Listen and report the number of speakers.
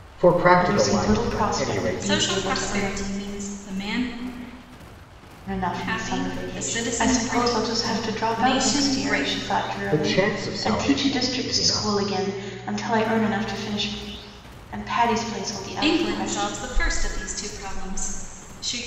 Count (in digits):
3